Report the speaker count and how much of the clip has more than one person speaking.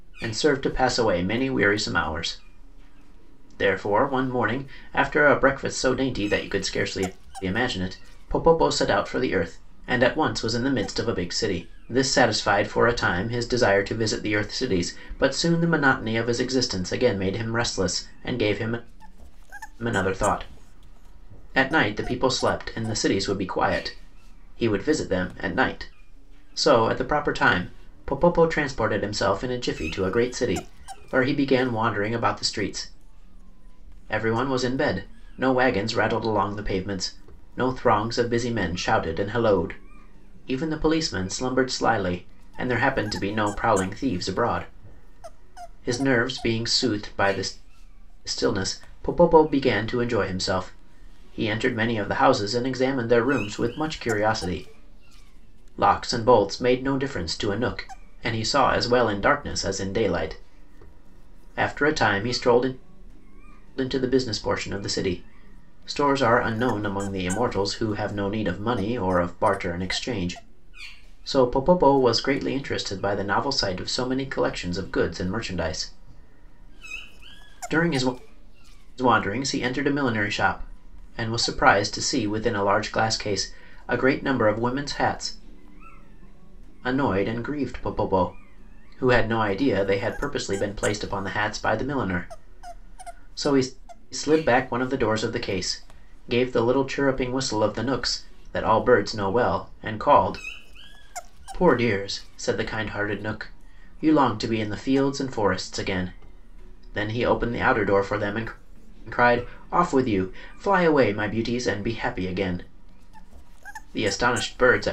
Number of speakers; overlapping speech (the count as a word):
one, no overlap